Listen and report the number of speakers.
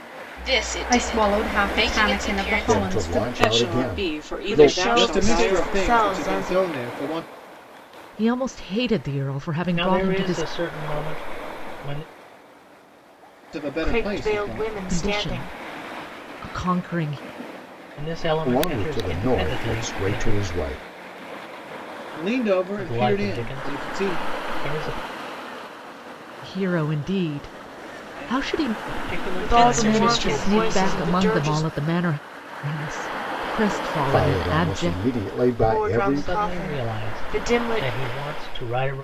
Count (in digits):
8